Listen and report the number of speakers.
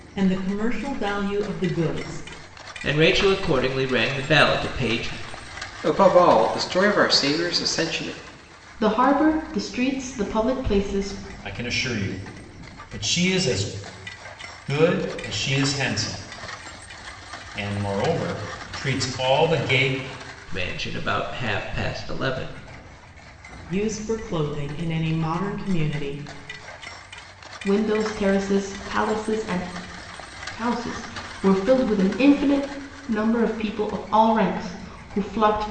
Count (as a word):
five